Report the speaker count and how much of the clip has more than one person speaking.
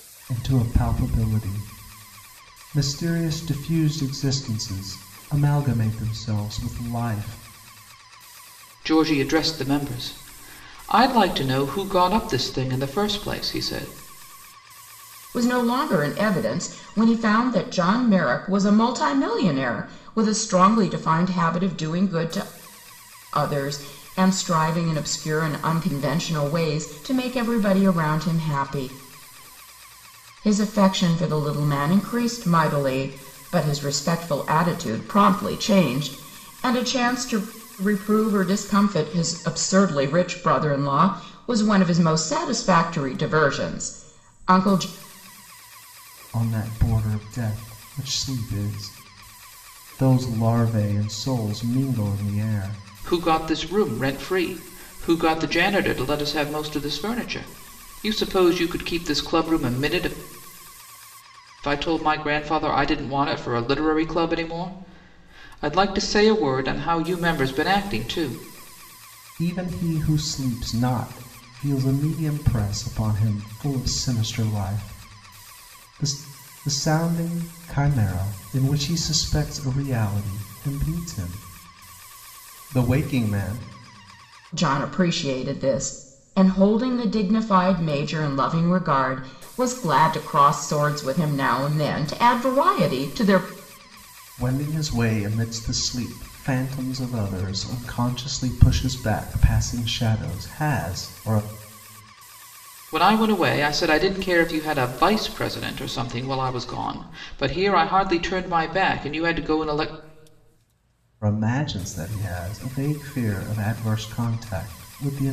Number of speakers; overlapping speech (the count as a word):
three, no overlap